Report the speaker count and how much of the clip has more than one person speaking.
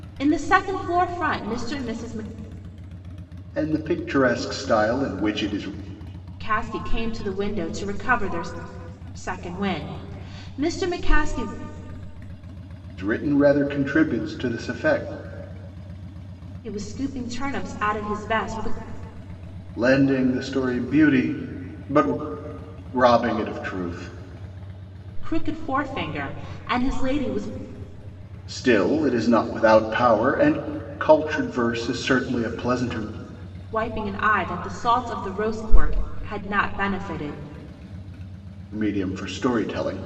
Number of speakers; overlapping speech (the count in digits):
2, no overlap